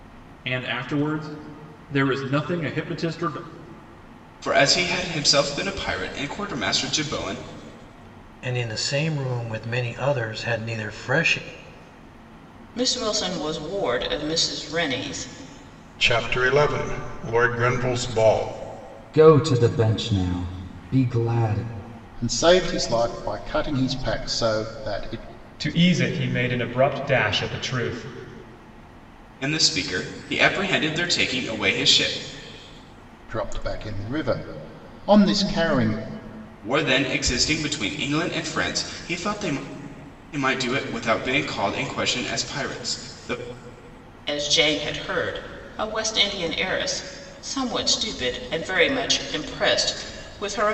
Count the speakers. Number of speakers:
8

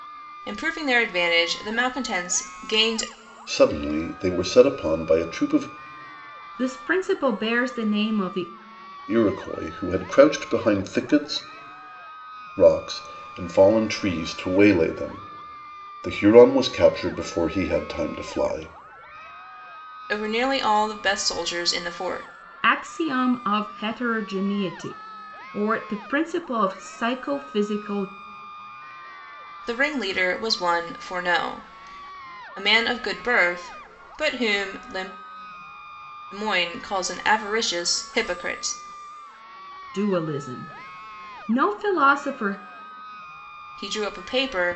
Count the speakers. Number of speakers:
3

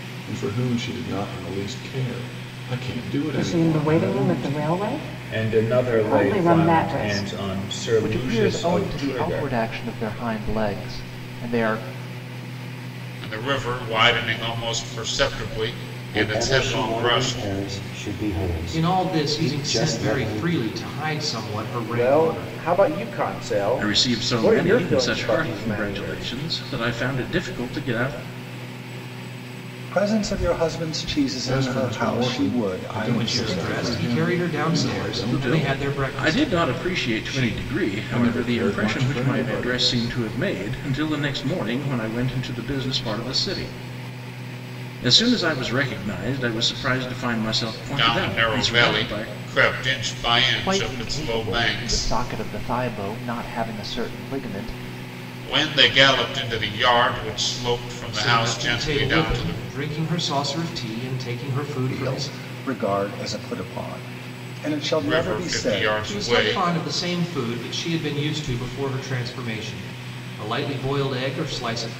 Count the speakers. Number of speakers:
10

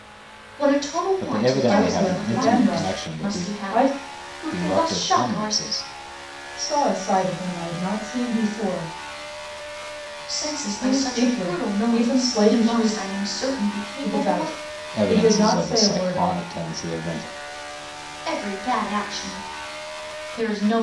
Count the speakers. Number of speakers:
3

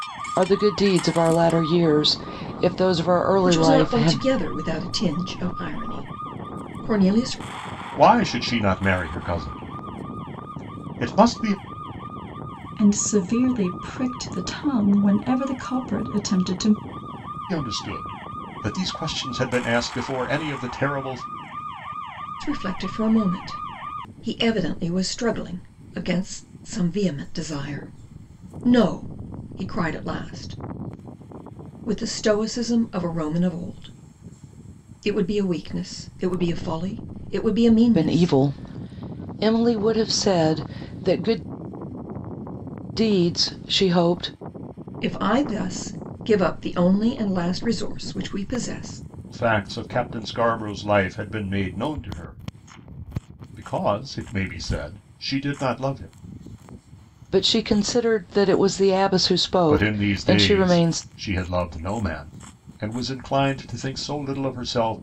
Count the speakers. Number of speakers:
4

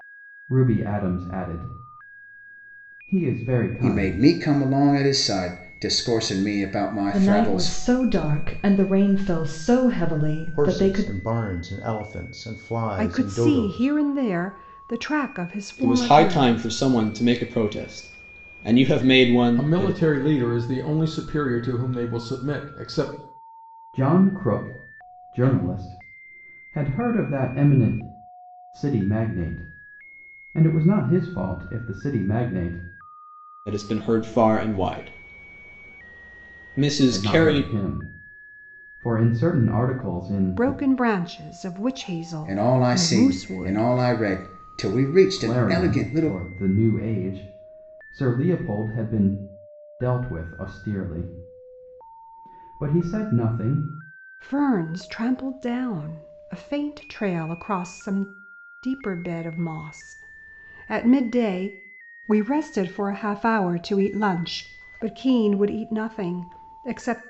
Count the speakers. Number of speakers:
7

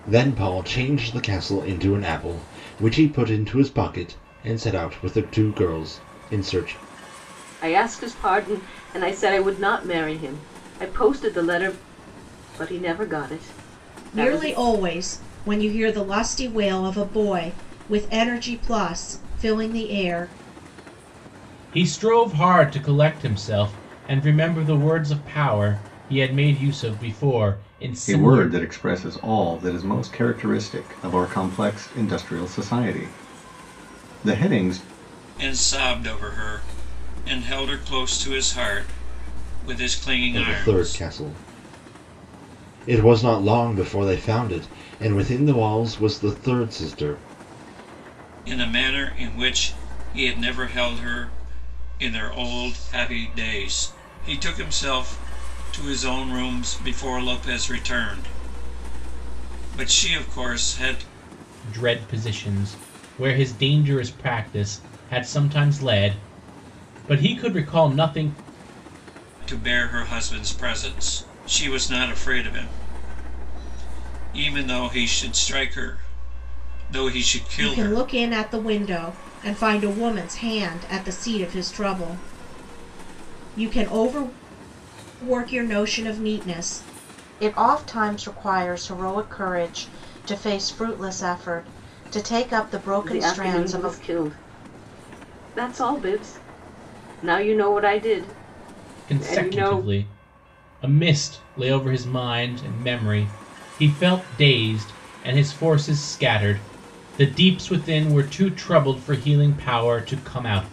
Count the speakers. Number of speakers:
6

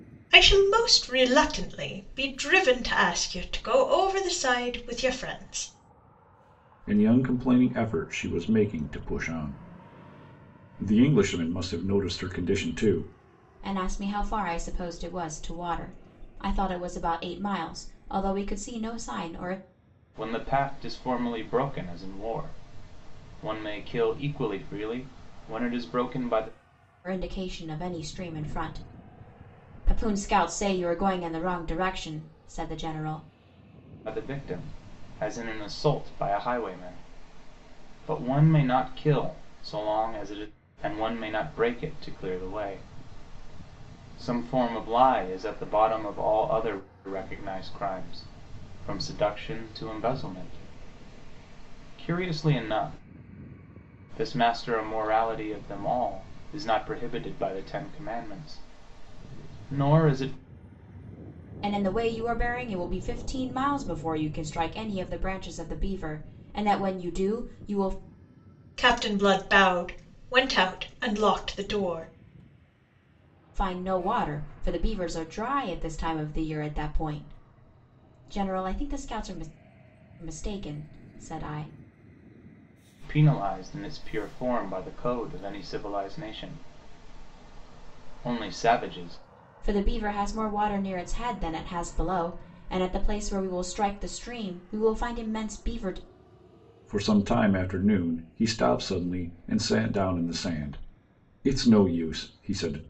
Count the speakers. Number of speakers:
4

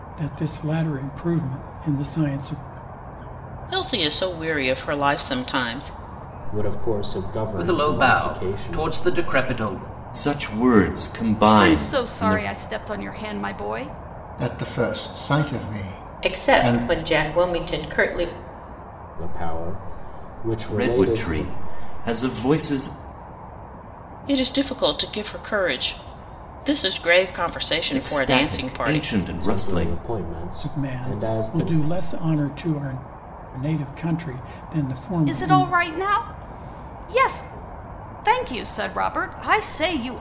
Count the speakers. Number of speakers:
8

